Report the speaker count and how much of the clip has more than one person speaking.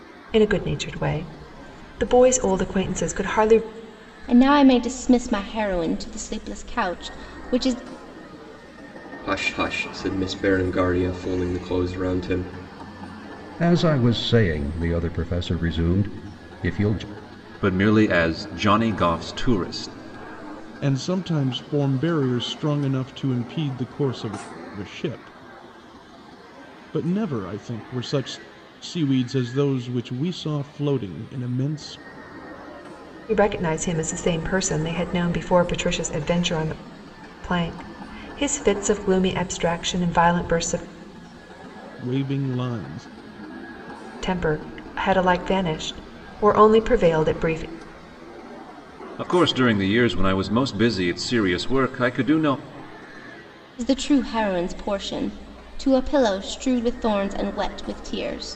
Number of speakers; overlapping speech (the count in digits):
6, no overlap